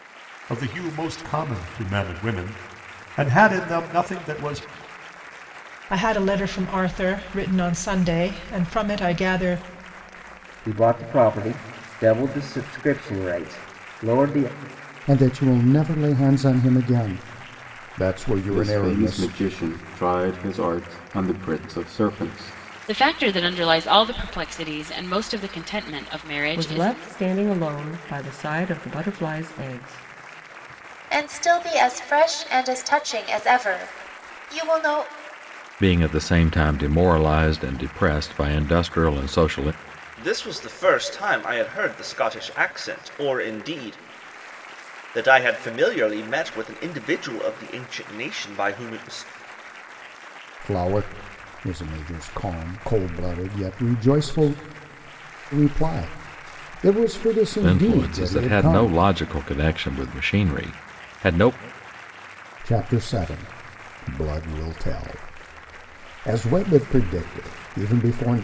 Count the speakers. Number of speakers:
ten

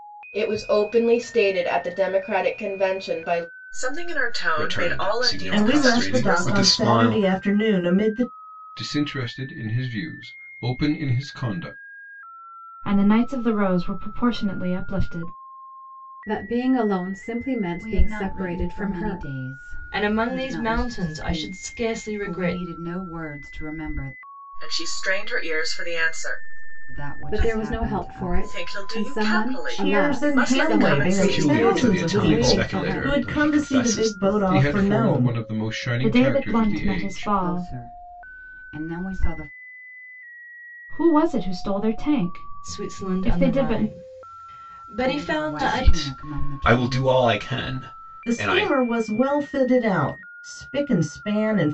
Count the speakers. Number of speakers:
nine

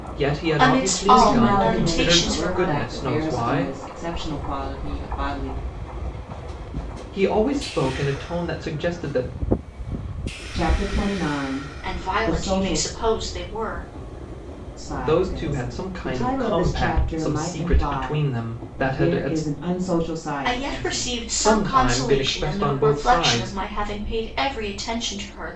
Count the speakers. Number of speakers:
three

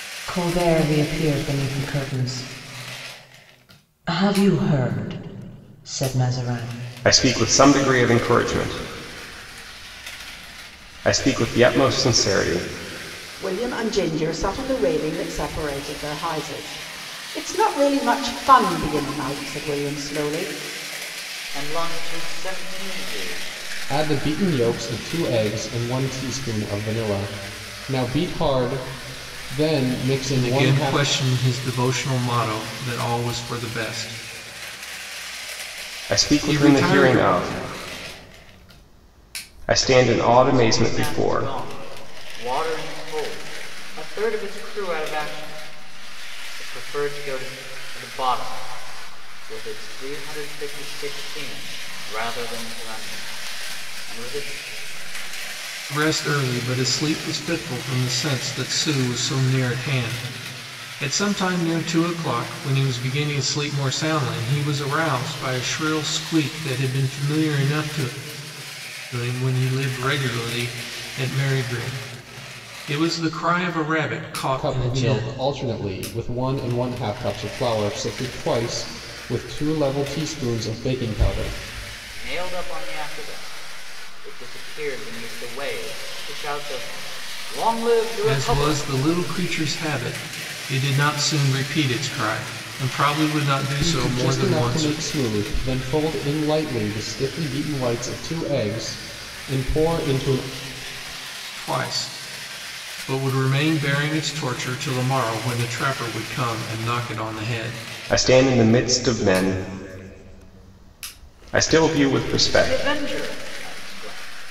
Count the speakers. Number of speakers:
six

